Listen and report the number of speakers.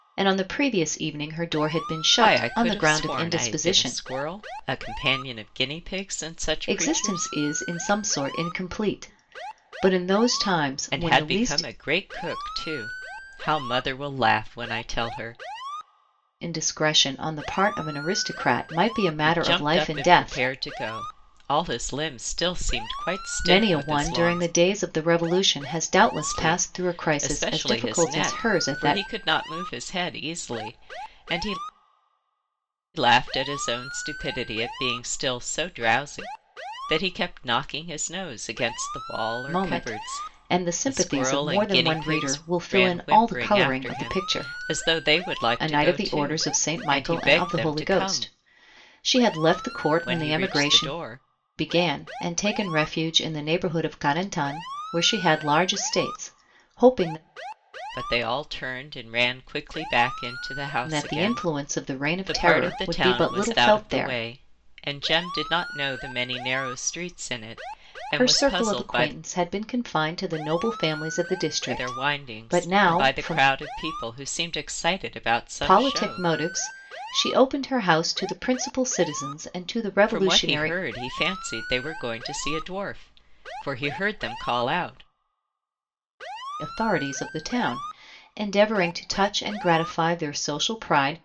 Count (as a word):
two